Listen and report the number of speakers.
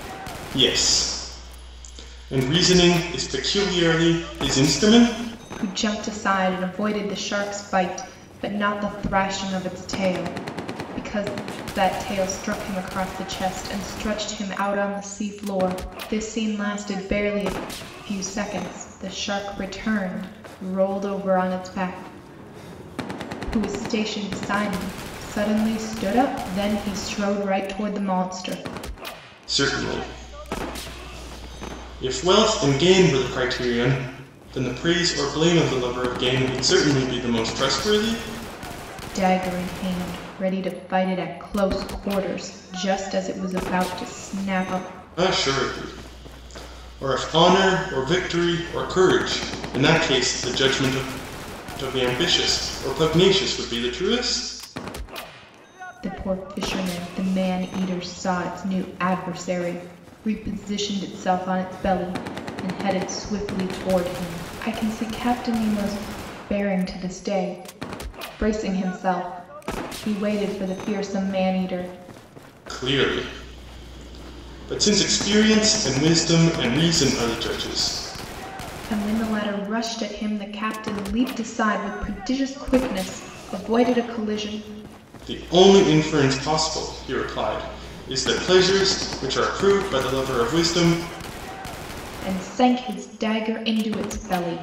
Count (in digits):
2